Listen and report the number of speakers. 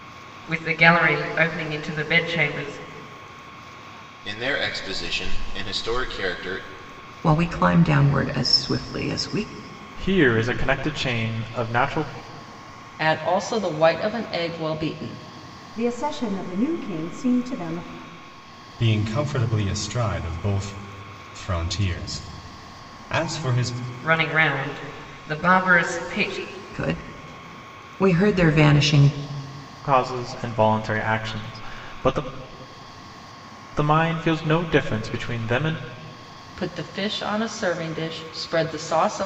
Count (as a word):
seven